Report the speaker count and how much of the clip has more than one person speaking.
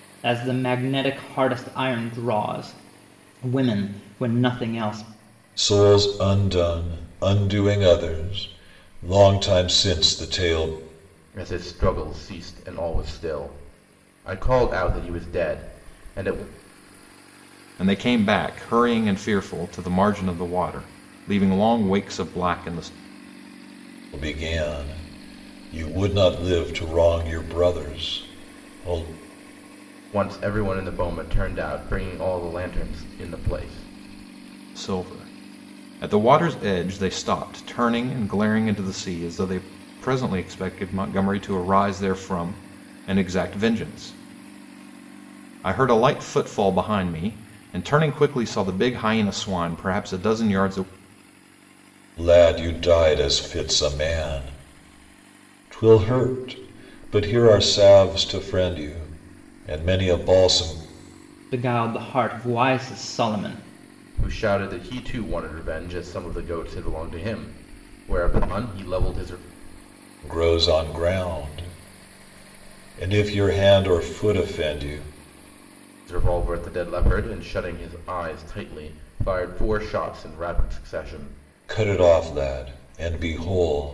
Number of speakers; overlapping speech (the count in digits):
4, no overlap